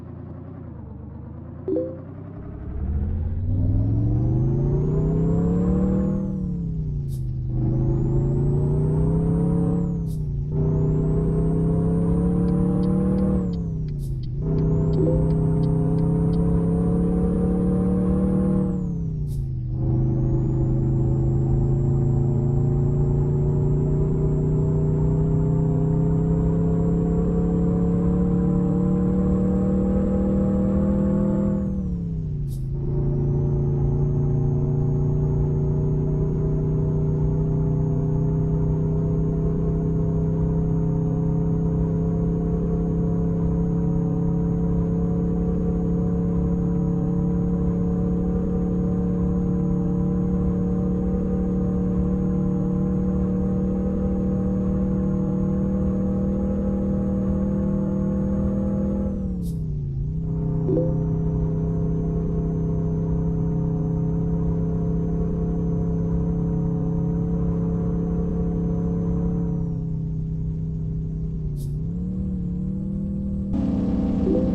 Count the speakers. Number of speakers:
zero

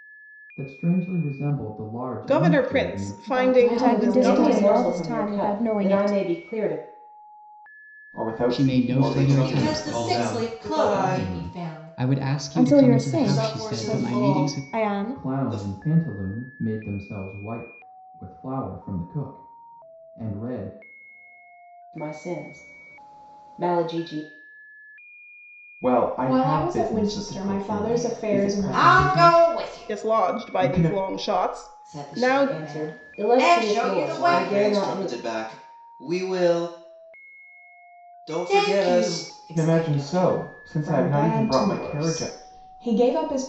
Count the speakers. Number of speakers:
nine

